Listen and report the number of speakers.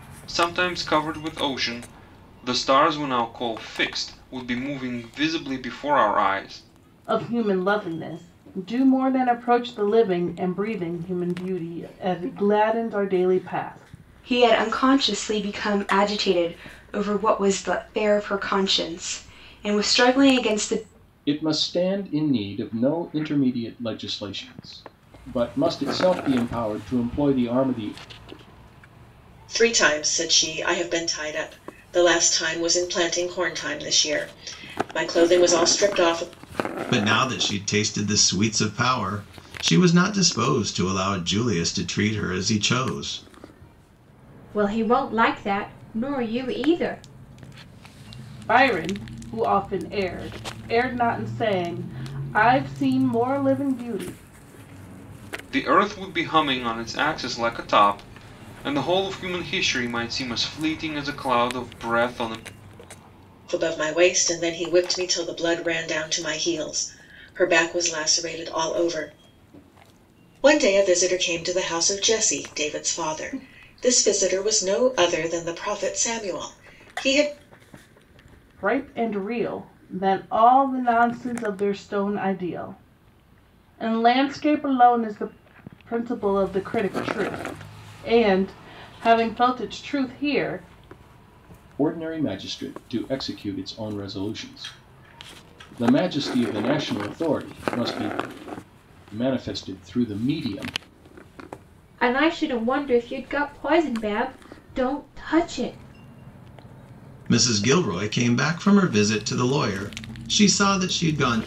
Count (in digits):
7